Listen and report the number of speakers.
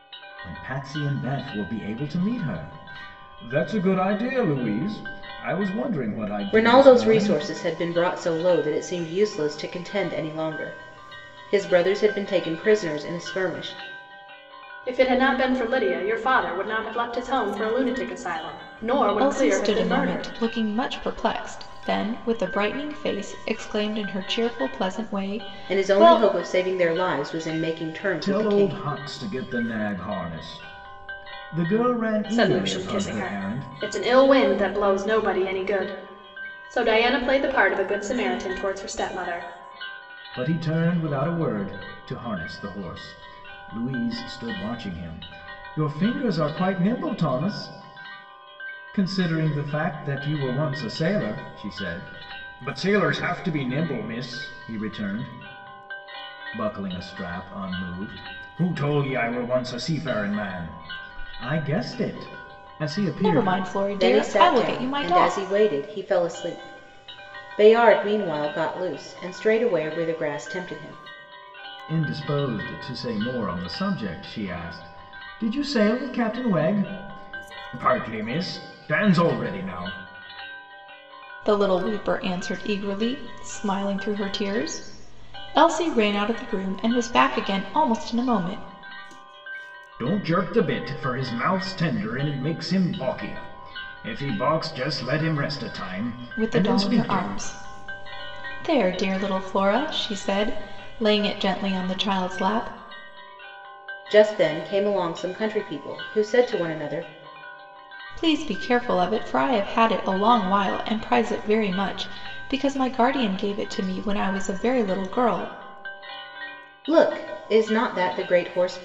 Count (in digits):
4